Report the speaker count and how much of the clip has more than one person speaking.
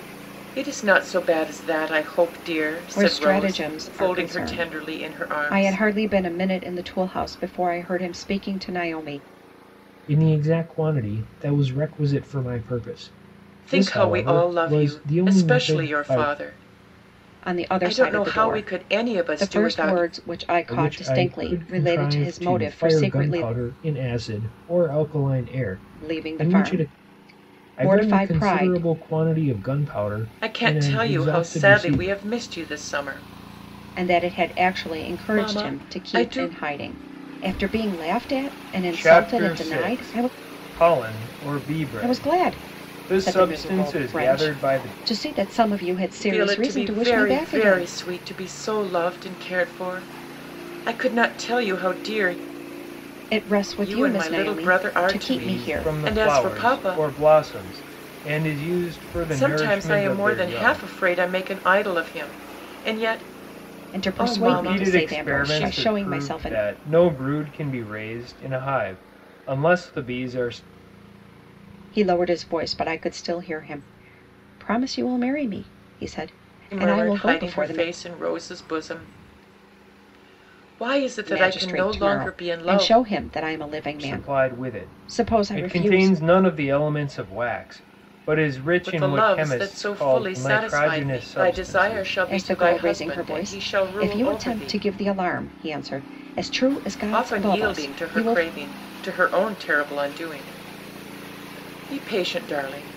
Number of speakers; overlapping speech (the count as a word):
three, about 42%